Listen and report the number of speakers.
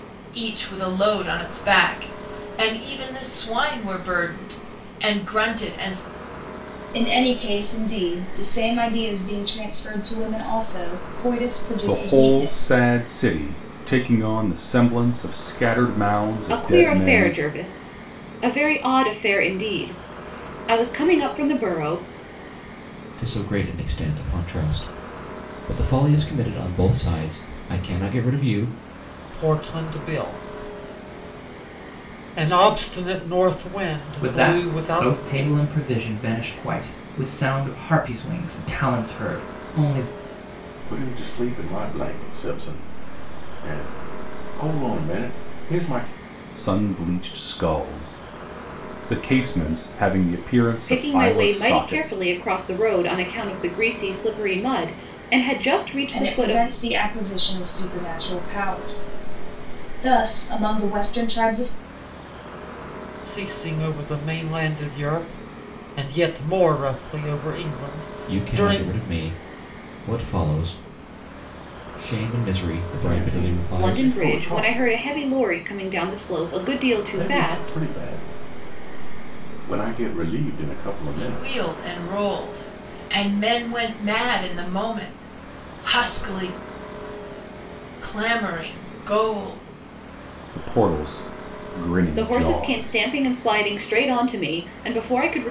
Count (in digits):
8